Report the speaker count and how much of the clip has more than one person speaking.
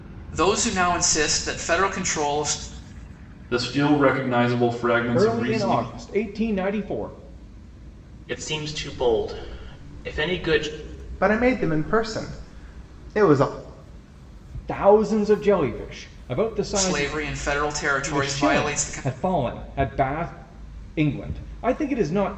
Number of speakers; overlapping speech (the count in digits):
5, about 9%